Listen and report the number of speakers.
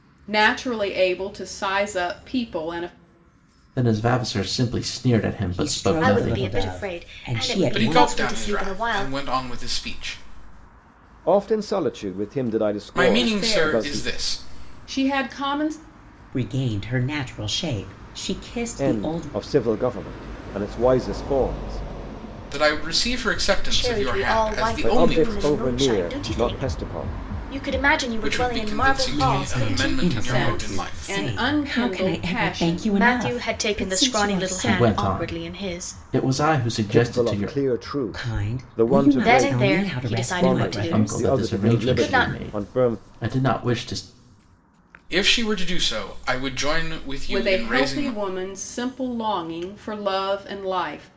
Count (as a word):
six